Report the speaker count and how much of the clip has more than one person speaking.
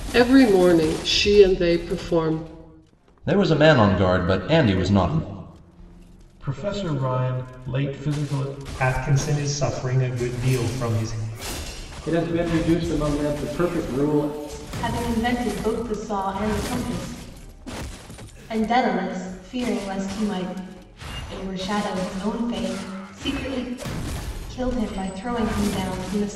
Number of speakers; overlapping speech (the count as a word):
six, no overlap